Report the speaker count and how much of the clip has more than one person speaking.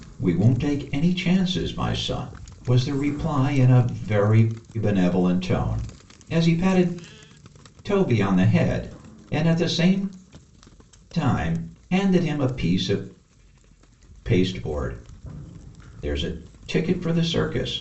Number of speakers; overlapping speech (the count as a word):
one, no overlap